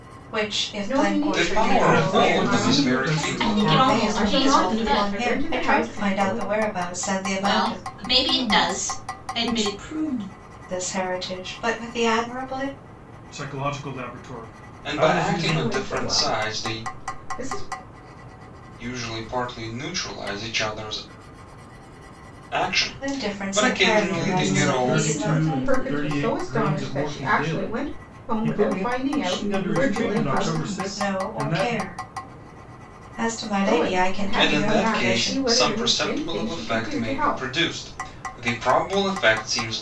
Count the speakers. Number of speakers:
six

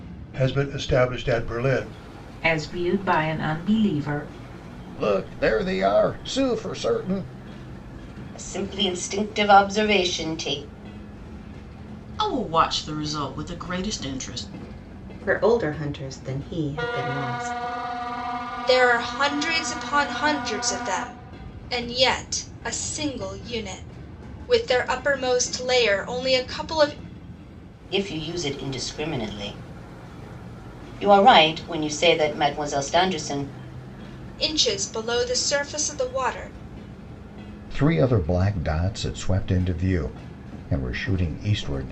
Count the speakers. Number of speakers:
seven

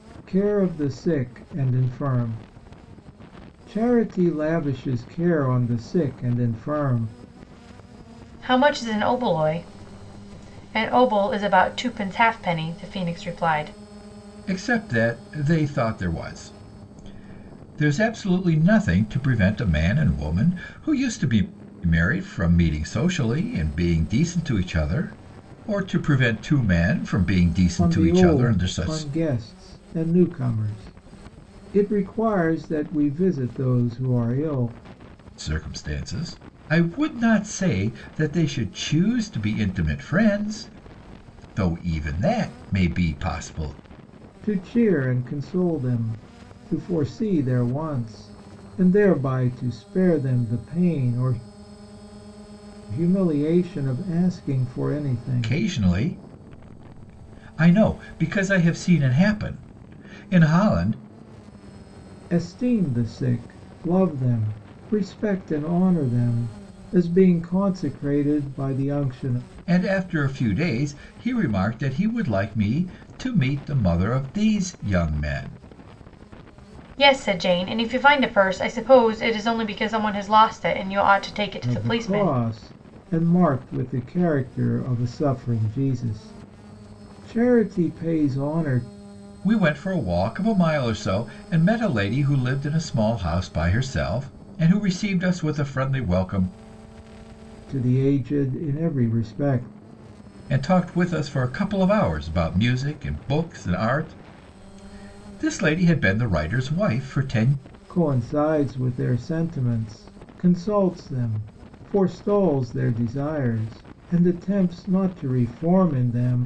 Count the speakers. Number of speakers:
three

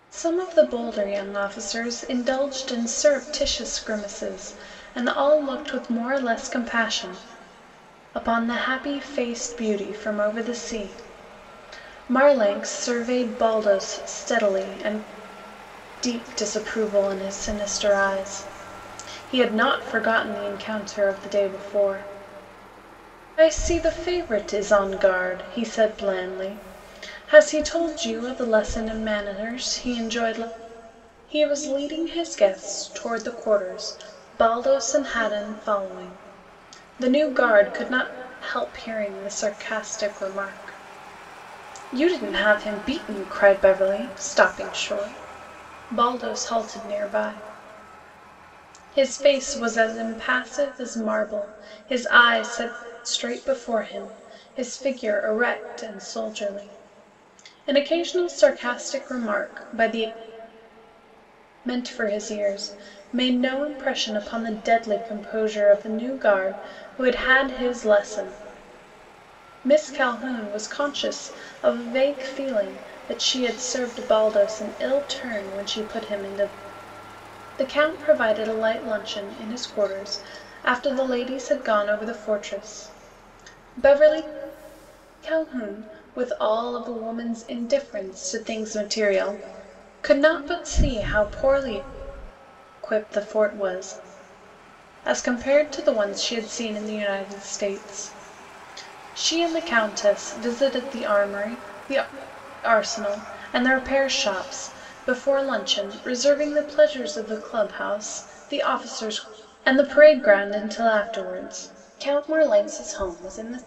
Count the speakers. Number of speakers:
one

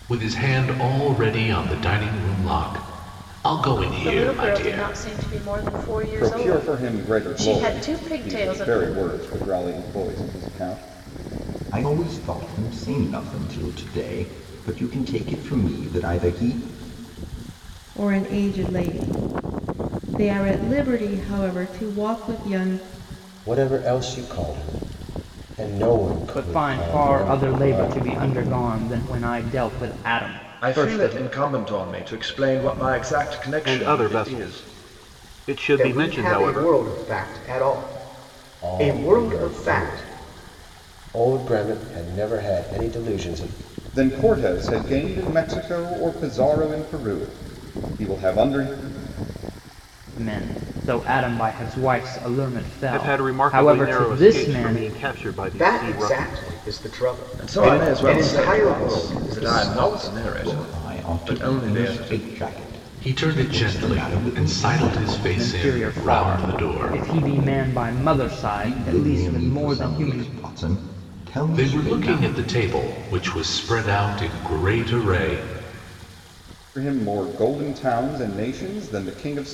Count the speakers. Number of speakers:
ten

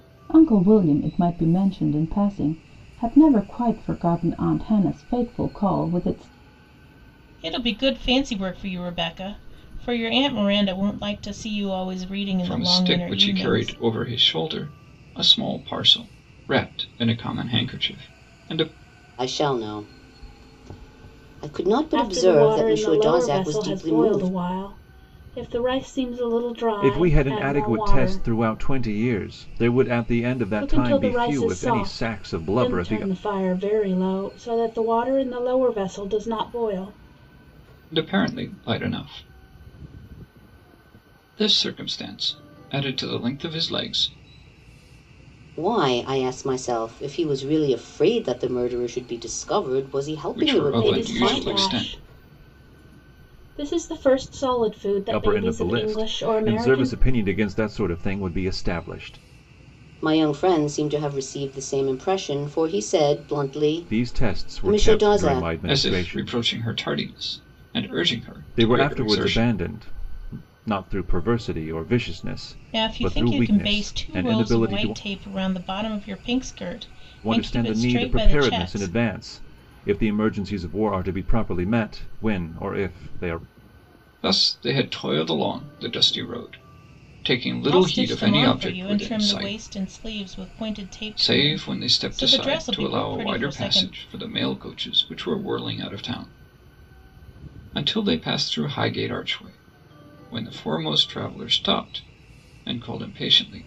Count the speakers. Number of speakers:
six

